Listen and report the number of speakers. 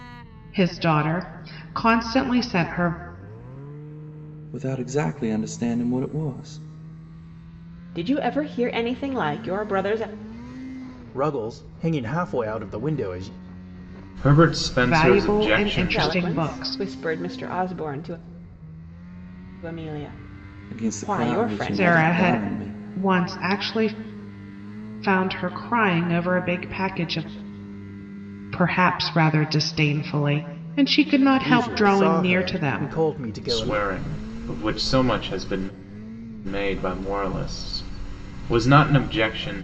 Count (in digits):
5